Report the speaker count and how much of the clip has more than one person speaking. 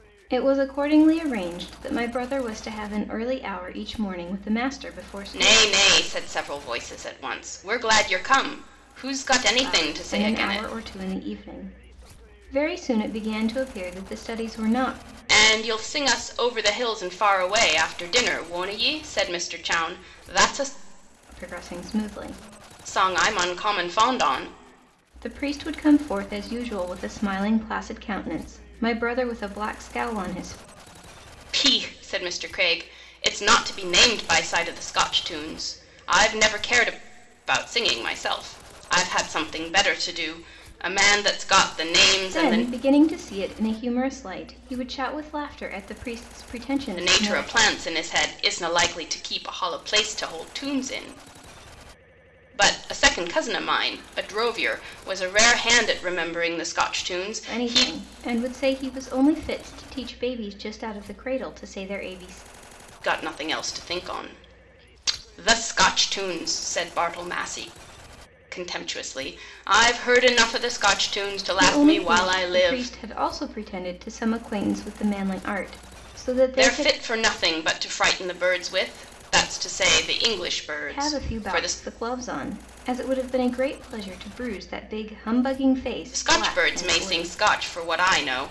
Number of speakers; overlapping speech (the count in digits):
2, about 8%